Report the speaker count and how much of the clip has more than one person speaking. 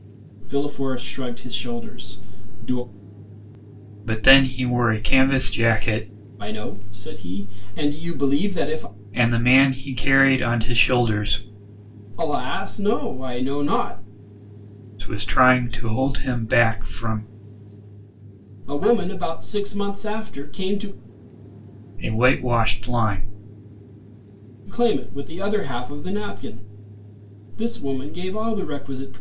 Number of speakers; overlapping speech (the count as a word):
two, no overlap